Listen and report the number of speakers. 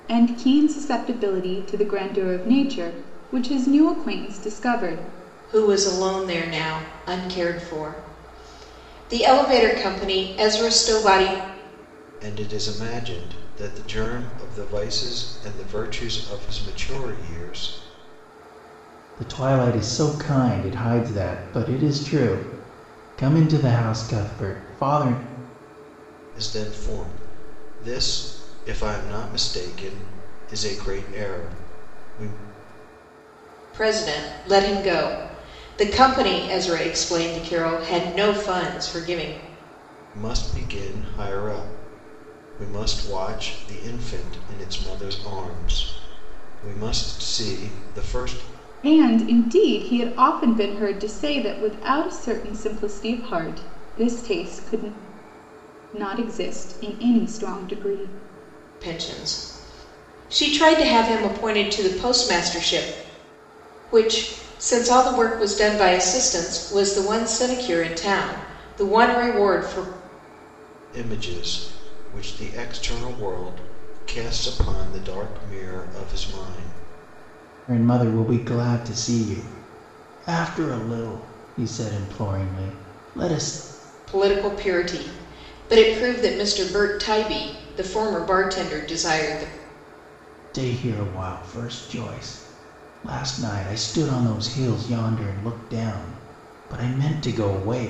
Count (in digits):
4